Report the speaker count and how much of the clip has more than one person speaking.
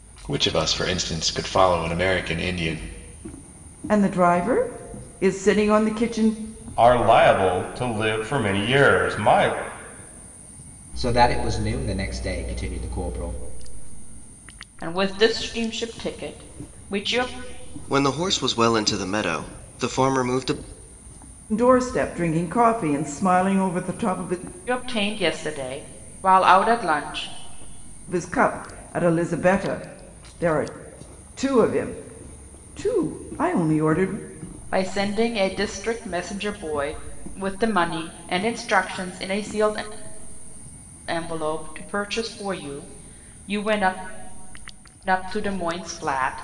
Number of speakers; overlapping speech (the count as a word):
six, no overlap